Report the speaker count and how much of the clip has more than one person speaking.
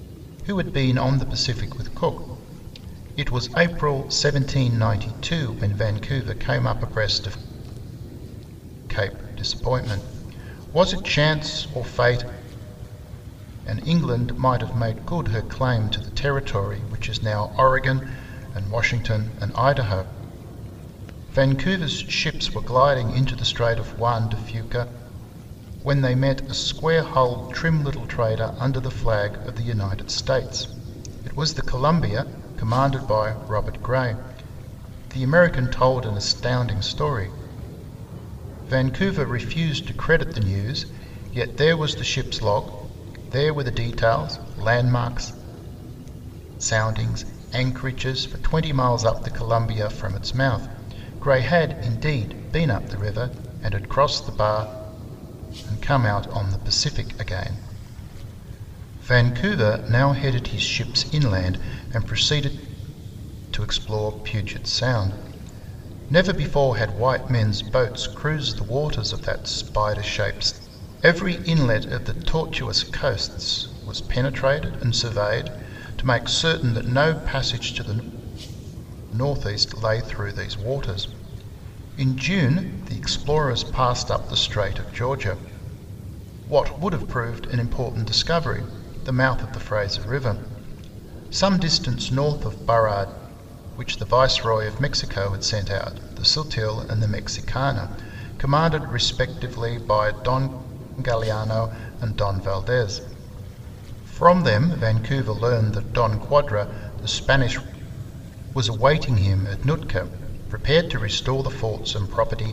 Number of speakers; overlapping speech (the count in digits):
1, no overlap